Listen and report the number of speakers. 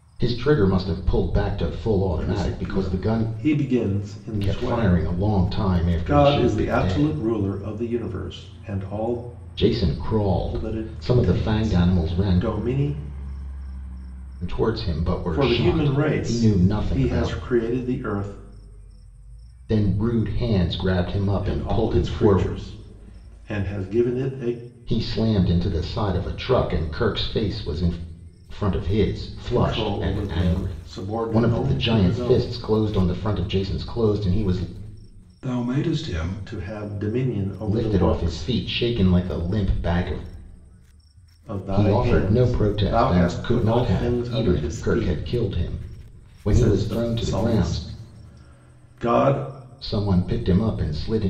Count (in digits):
2